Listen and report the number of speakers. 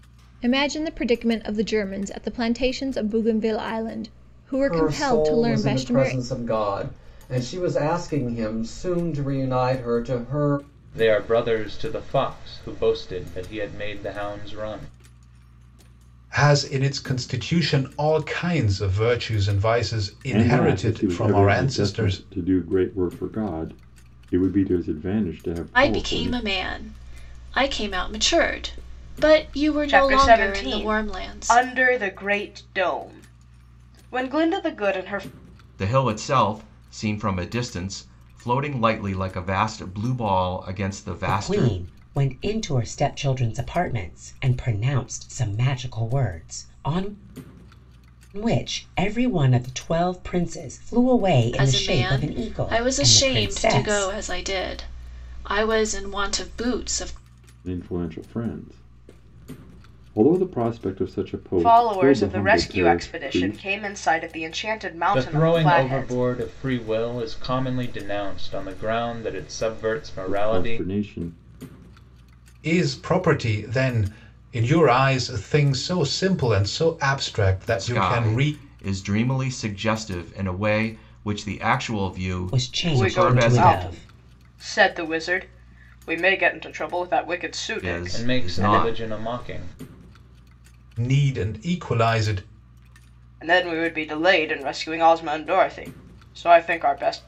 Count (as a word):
nine